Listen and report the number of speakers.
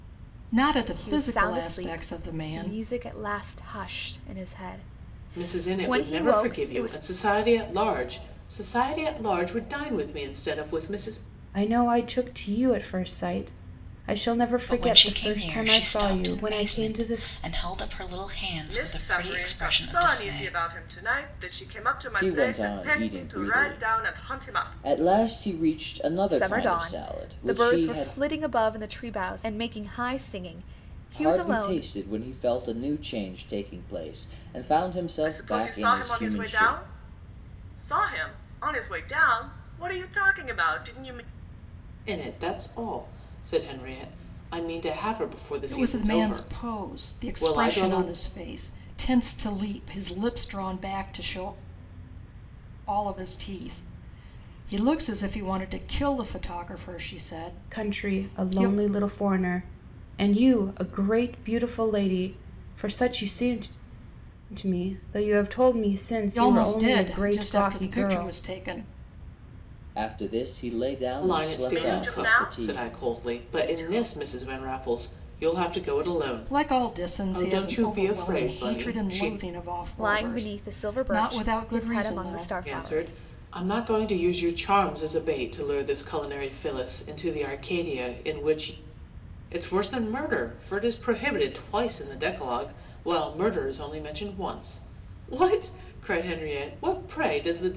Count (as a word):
seven